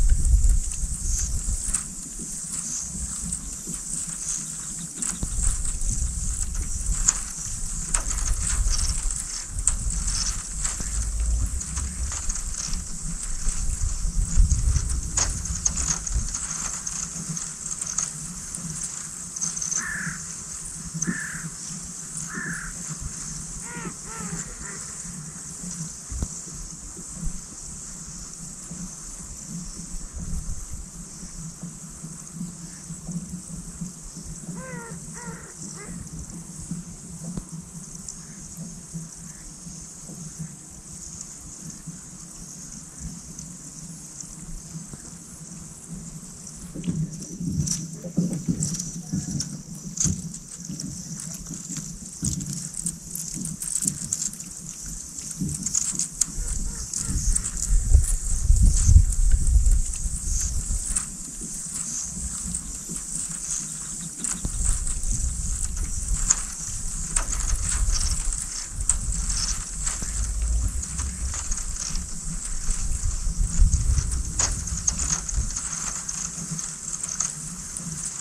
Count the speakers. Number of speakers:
0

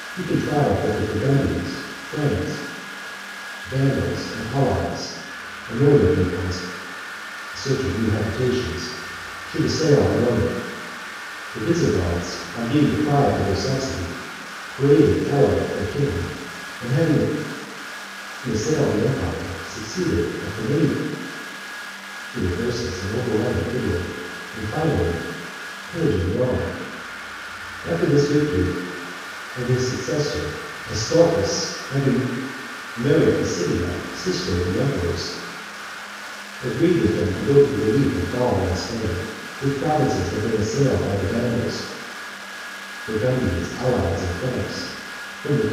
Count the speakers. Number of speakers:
1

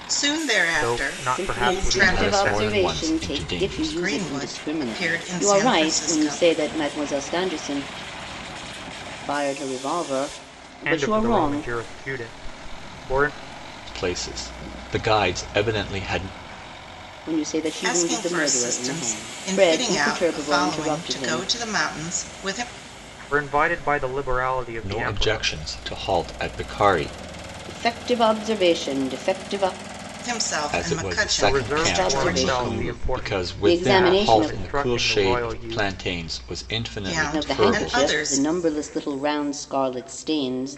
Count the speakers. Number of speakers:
4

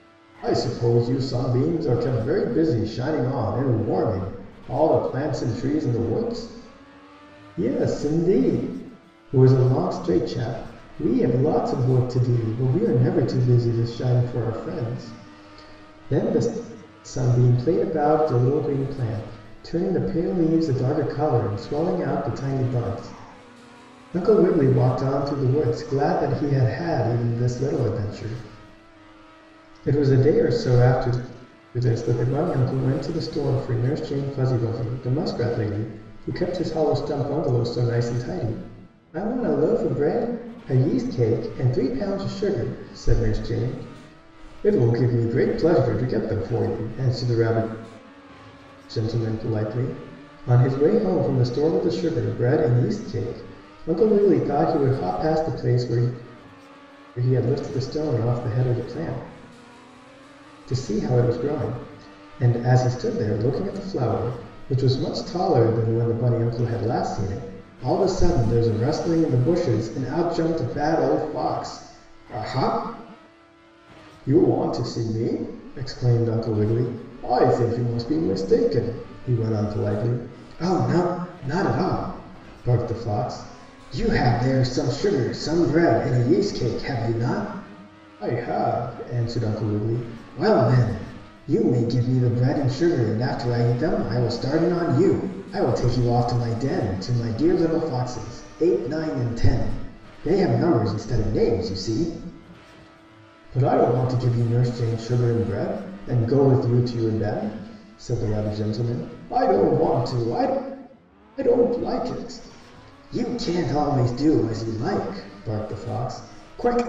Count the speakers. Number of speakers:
1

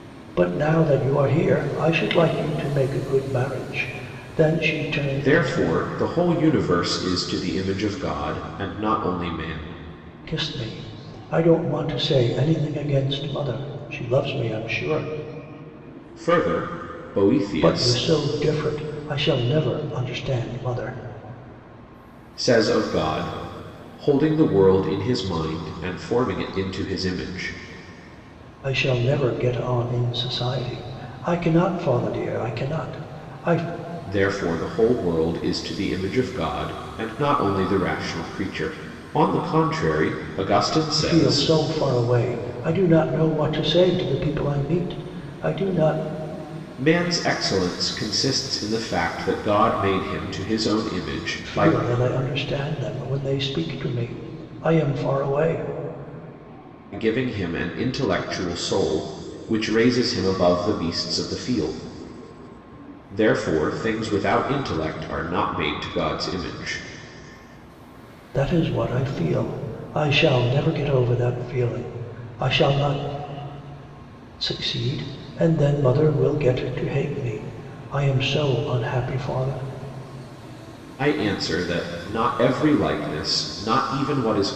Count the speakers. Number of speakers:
2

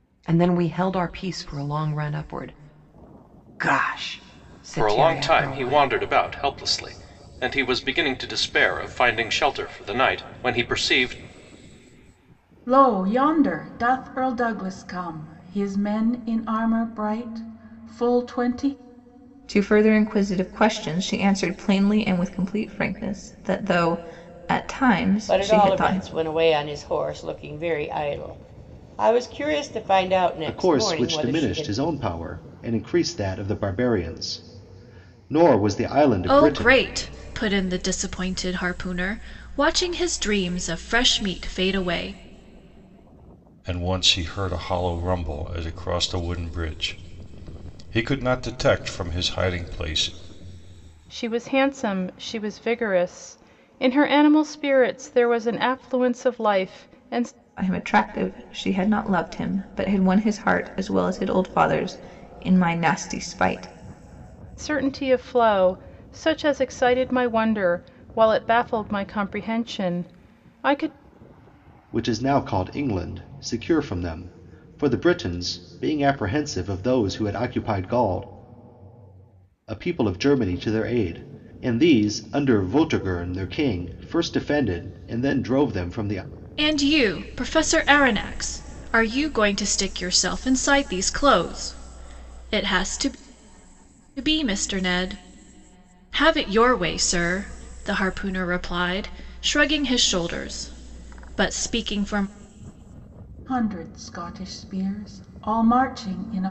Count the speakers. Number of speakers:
9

